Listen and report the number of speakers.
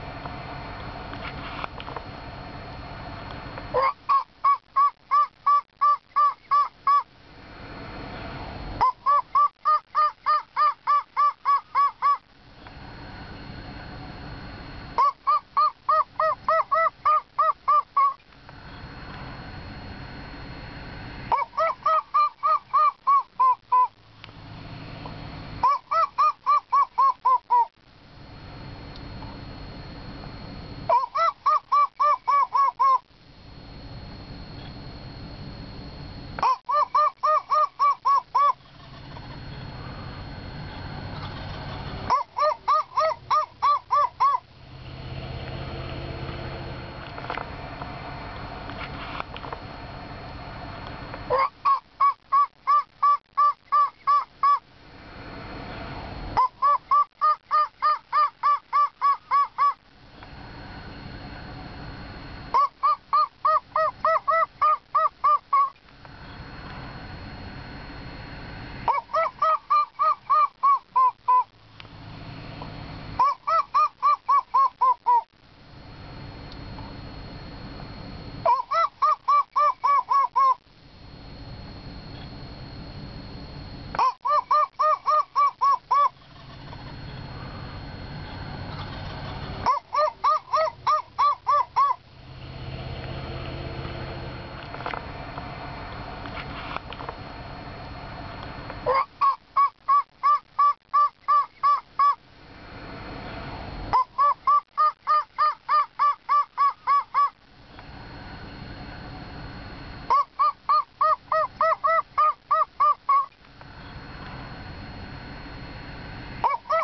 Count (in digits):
0